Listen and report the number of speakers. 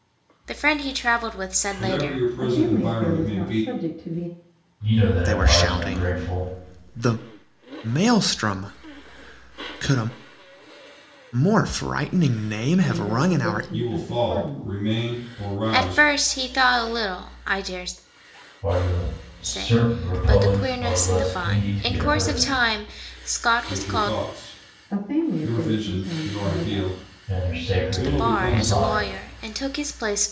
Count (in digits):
5